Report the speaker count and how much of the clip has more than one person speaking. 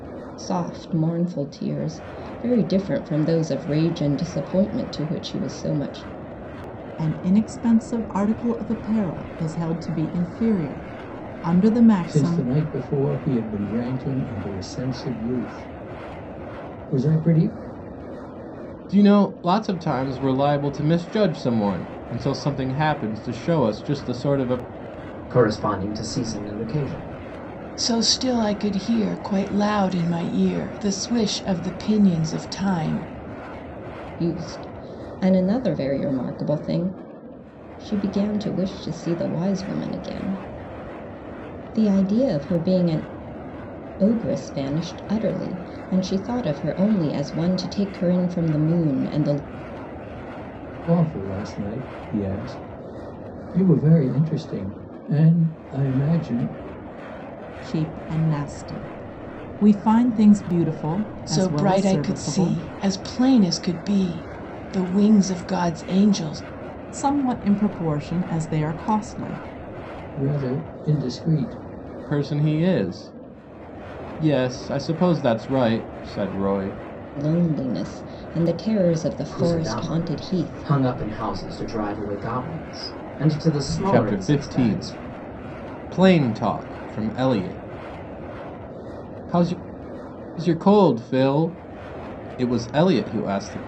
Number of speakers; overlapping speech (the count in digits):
6, about 5%